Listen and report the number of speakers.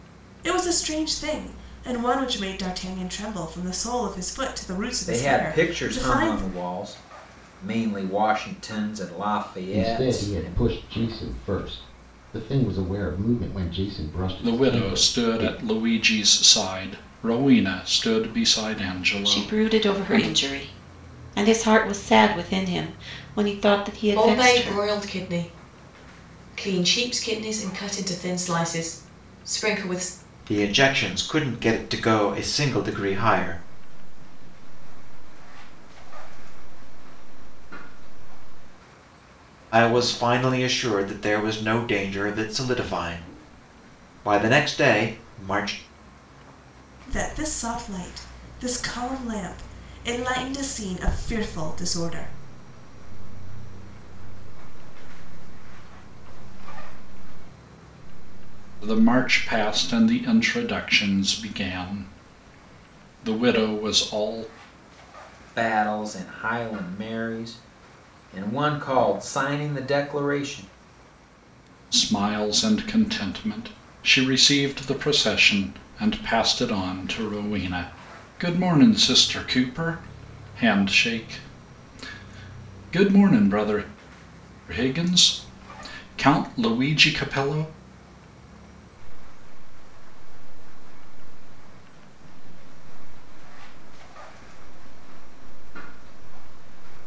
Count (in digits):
8